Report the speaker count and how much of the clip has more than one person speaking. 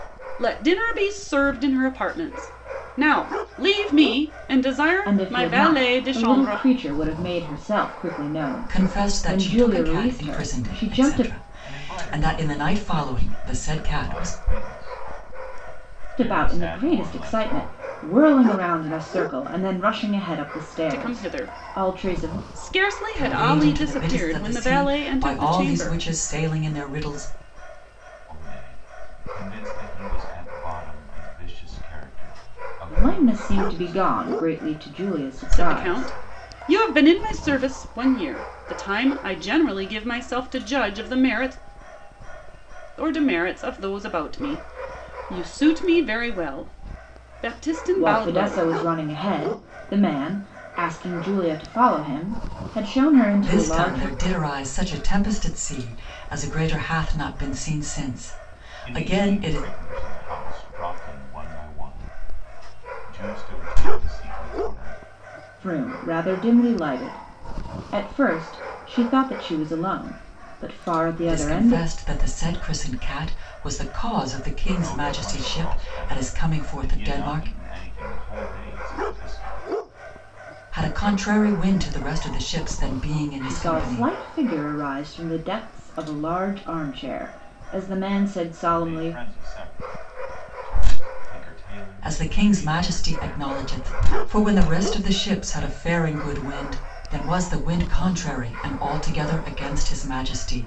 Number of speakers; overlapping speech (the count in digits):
4, about 25%